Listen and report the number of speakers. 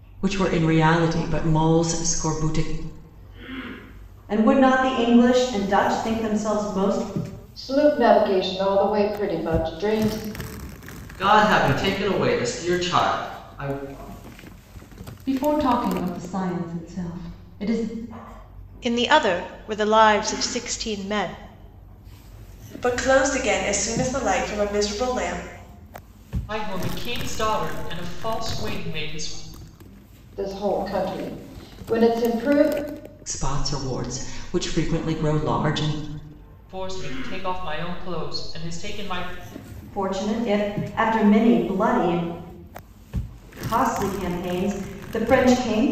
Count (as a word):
eight